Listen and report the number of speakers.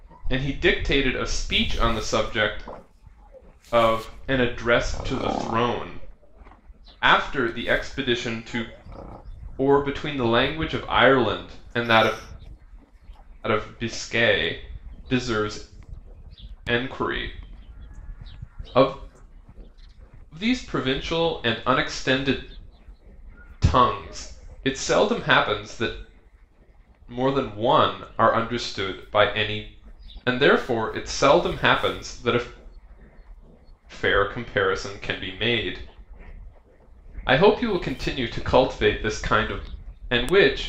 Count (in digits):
1